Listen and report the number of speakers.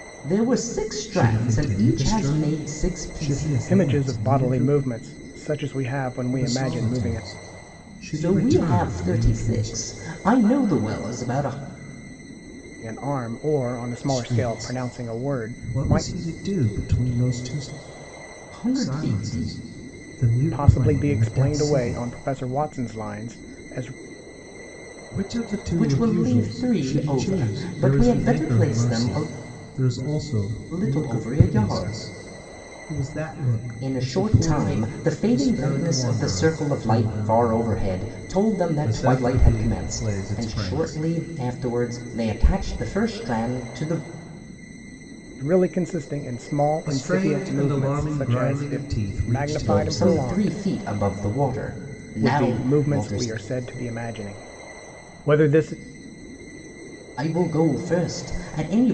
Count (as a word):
three